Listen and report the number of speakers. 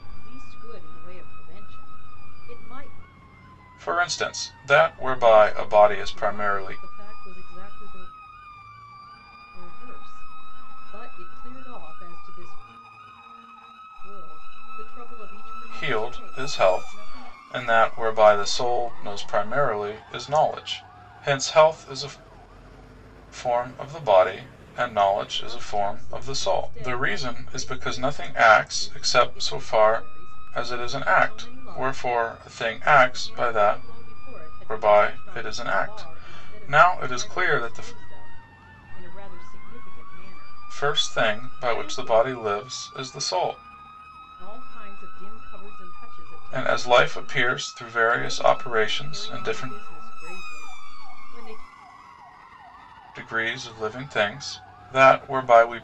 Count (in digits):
2